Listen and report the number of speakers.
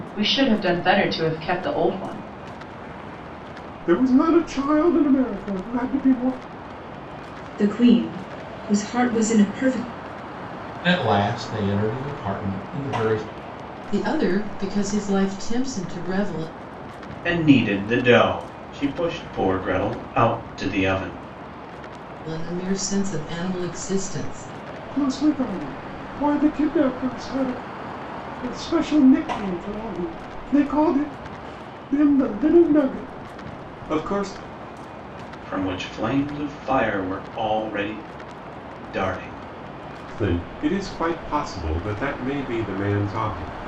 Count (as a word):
six